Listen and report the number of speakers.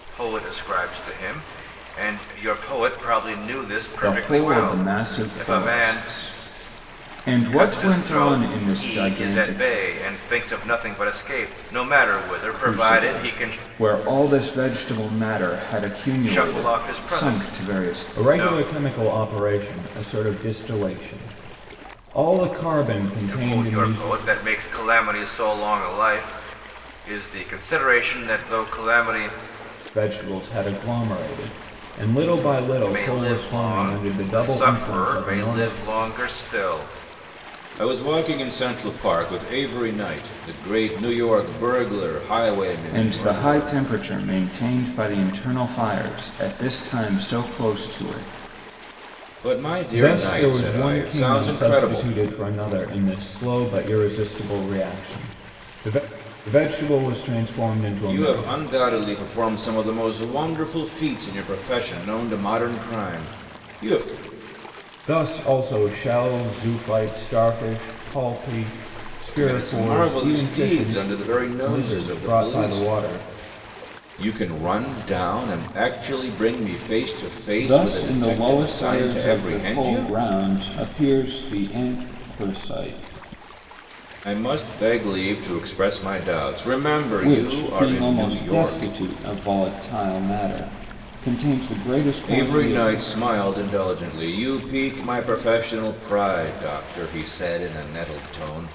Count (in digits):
2